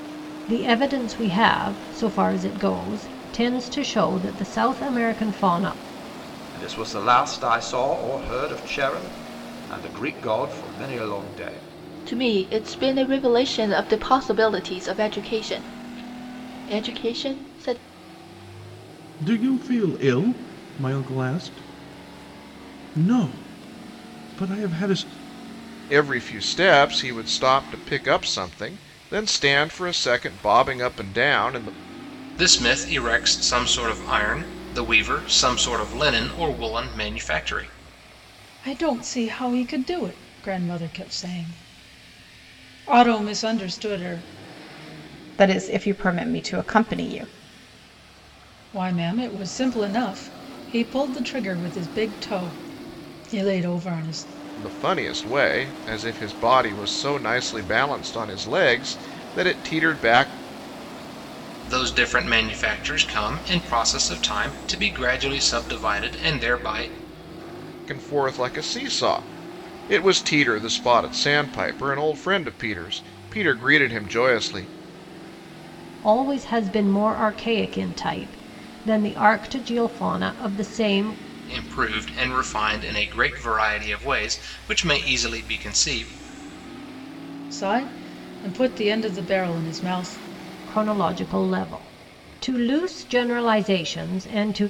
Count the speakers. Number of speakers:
8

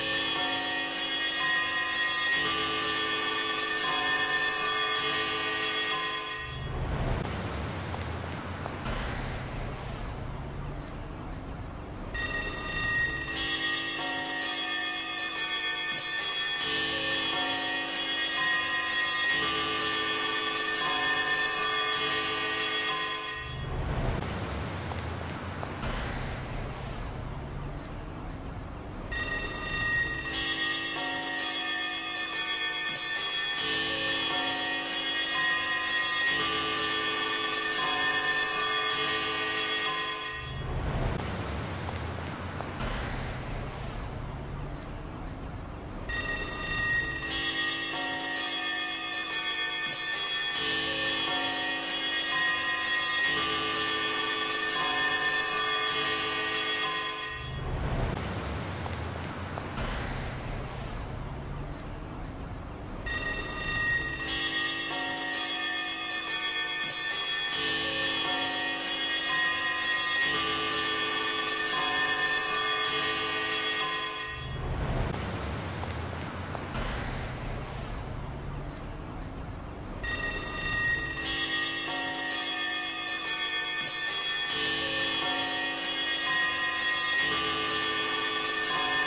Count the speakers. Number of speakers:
0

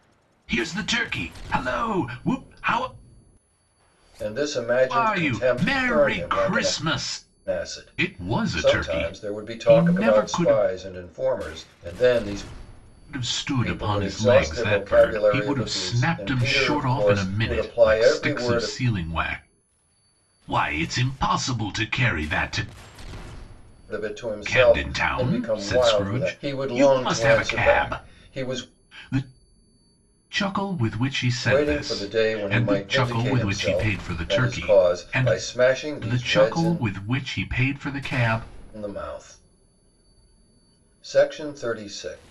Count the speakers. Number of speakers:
2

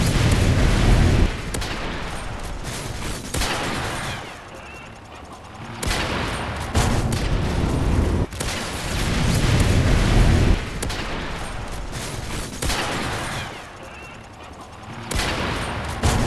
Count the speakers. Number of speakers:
0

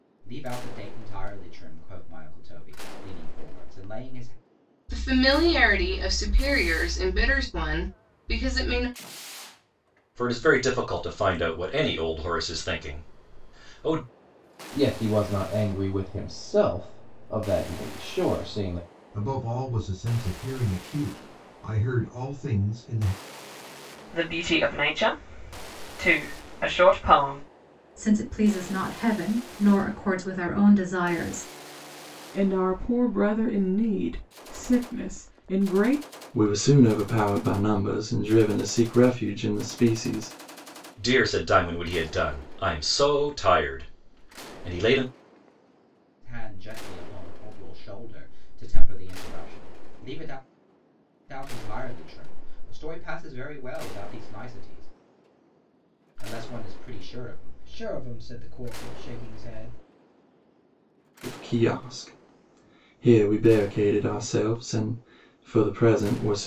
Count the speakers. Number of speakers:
9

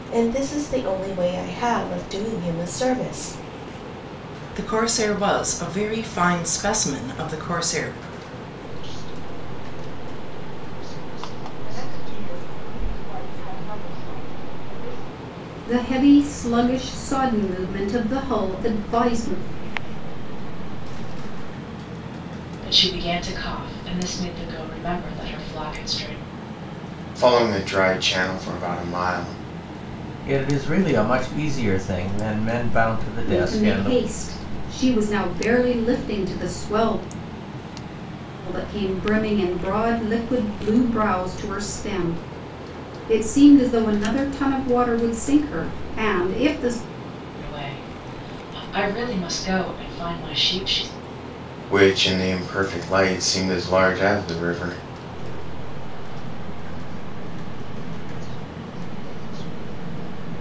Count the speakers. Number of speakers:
9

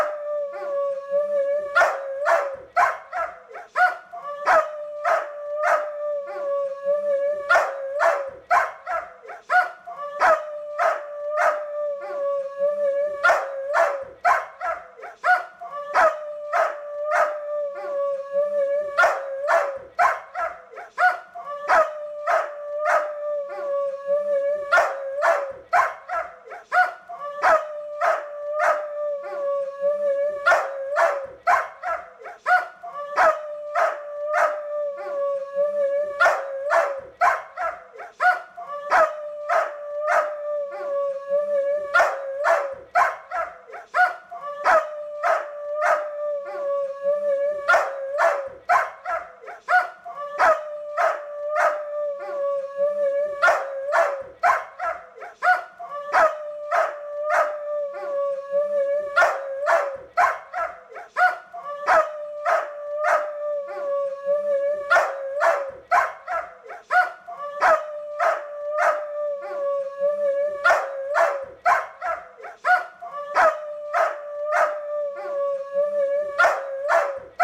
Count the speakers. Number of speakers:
0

